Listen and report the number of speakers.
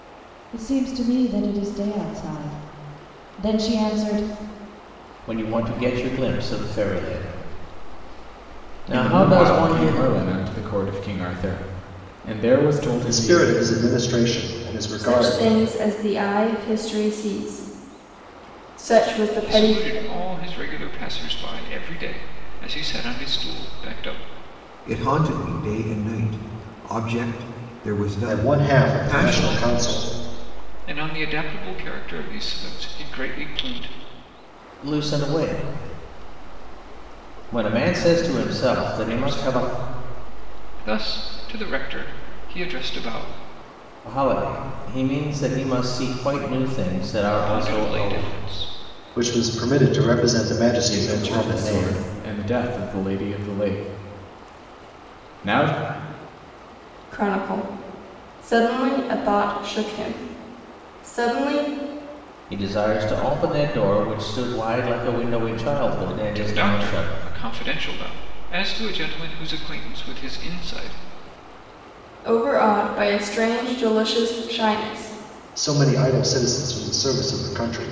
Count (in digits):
7